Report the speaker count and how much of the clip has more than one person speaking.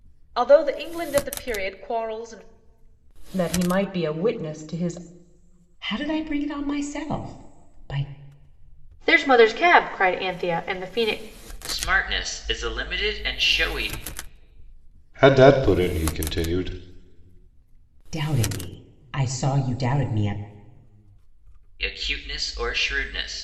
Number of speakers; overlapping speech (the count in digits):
6, no overlap